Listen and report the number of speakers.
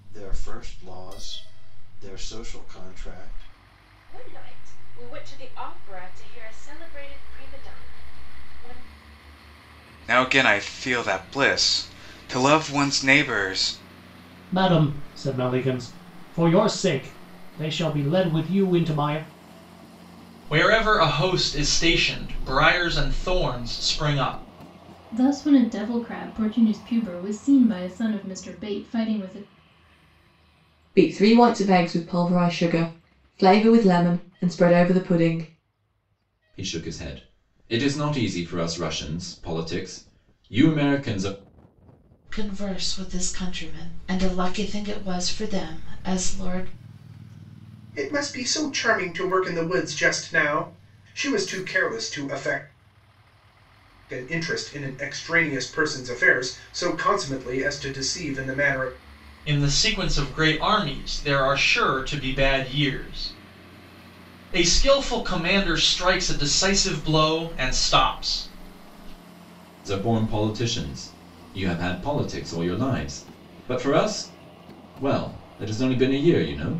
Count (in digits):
10